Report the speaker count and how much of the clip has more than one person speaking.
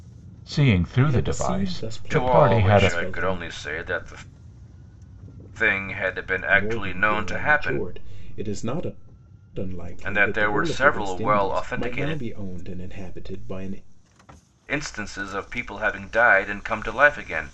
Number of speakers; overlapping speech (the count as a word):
three, about 34%